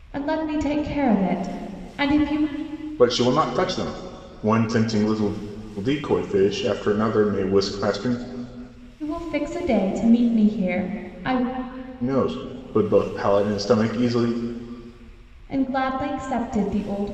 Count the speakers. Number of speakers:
two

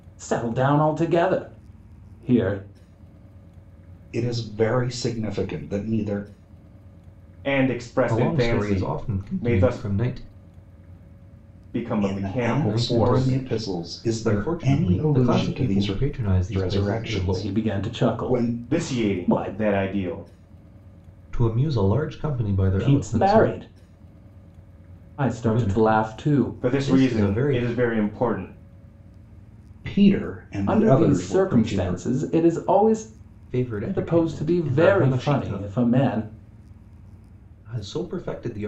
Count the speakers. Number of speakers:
four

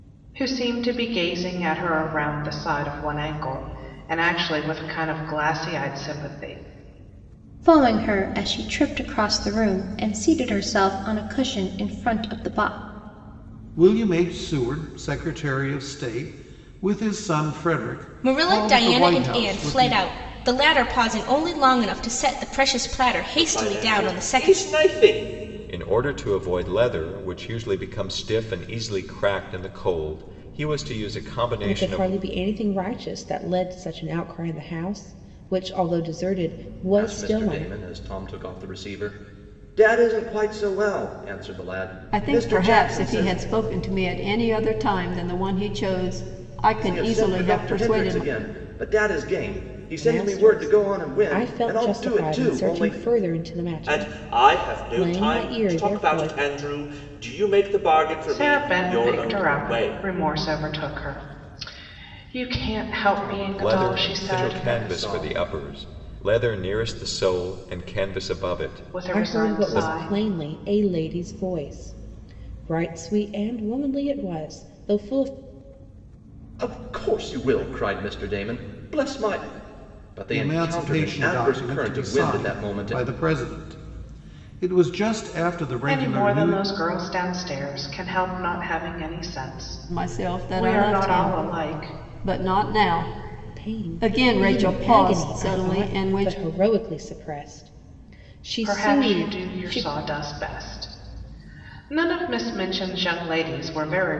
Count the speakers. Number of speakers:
nine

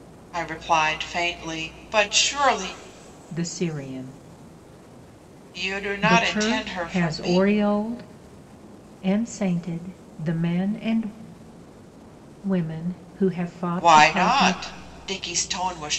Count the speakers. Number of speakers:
two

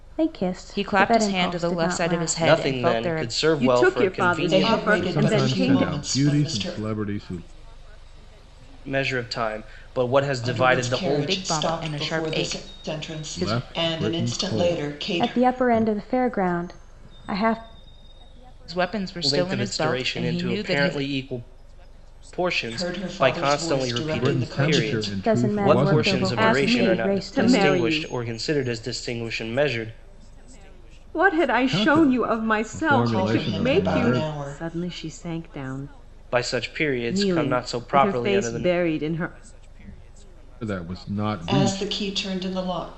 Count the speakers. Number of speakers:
six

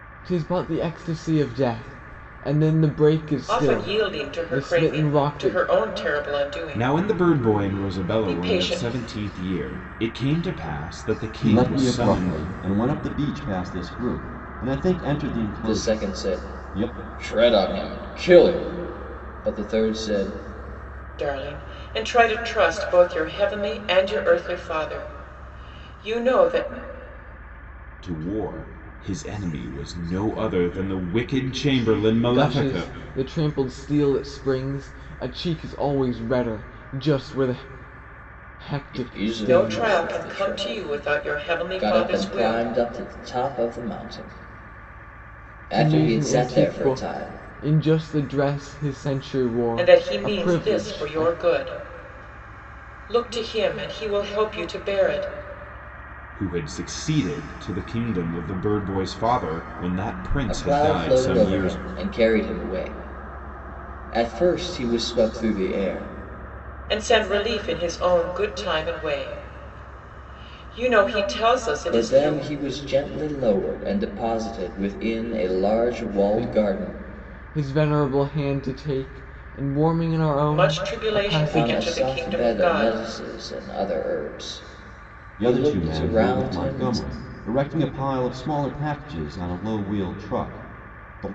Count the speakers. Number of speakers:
five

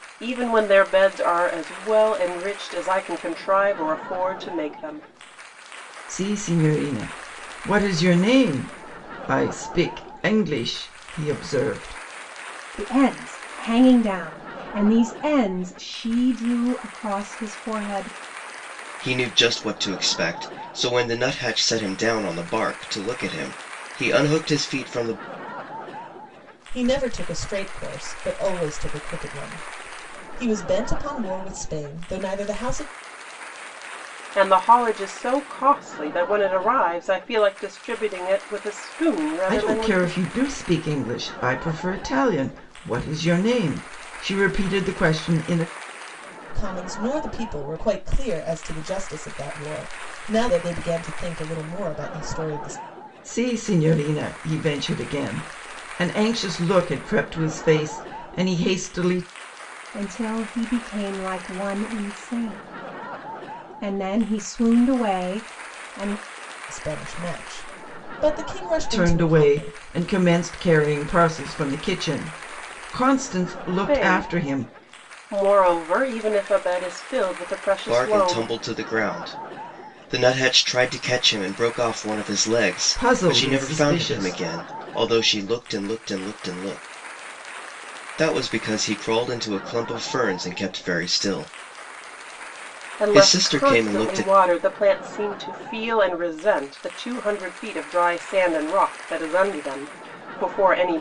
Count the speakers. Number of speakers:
five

